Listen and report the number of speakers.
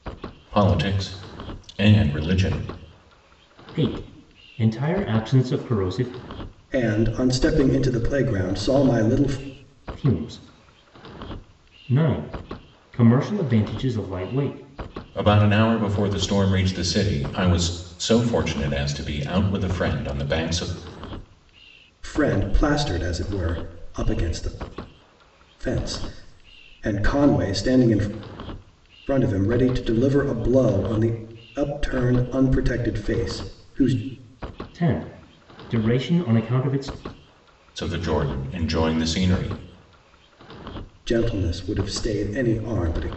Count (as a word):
three